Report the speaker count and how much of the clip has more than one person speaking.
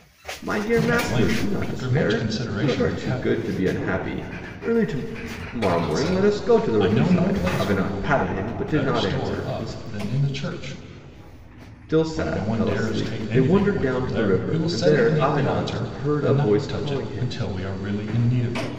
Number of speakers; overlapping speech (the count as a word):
two, about 60%